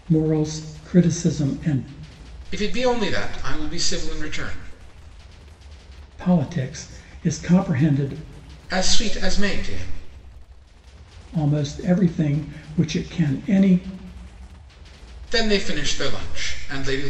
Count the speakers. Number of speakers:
2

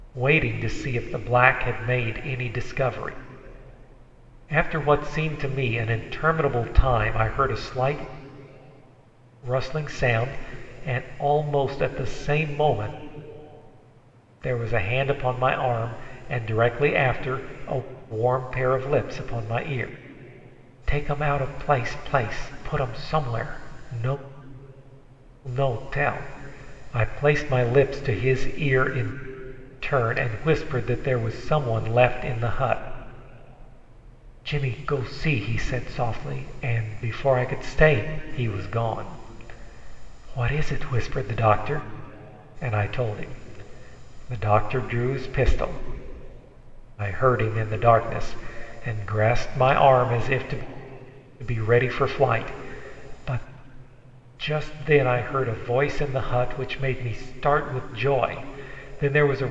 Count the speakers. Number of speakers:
1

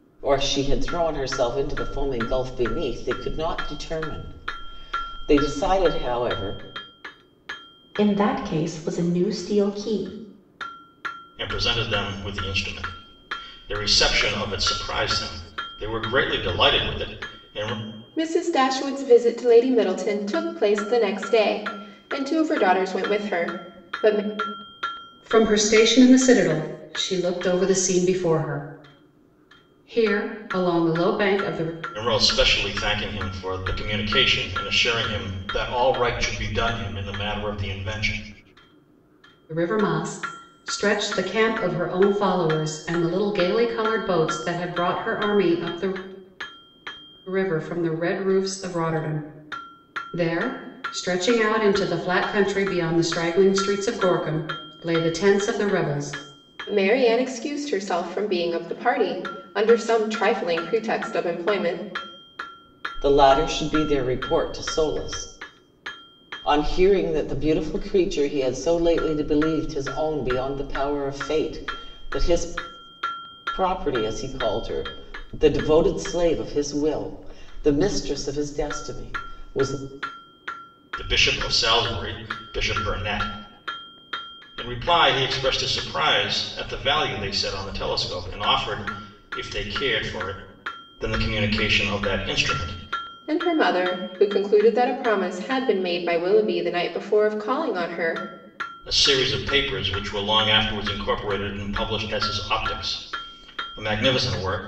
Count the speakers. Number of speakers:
5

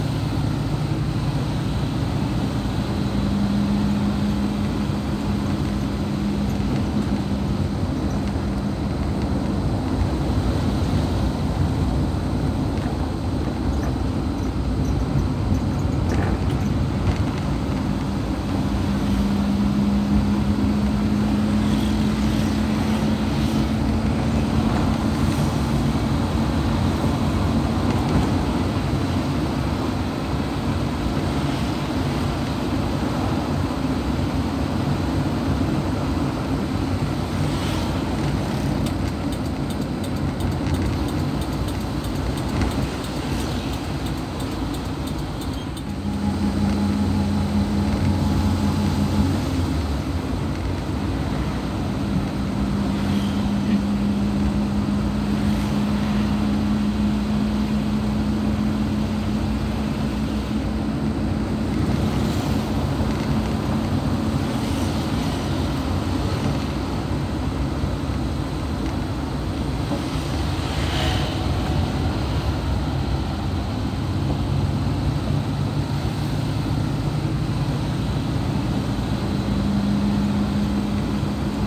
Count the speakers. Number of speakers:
0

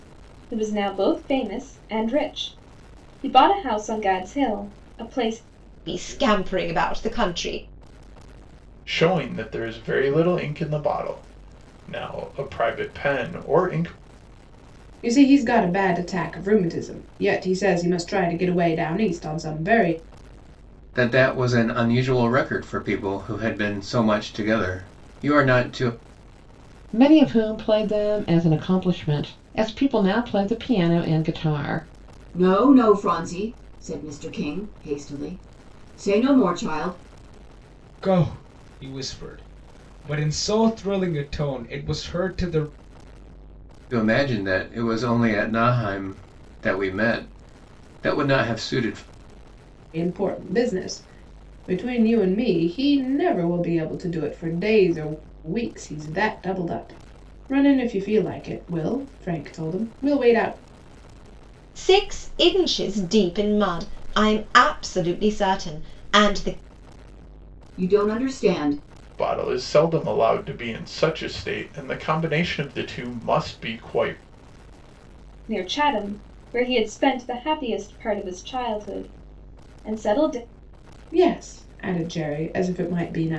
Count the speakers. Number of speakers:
8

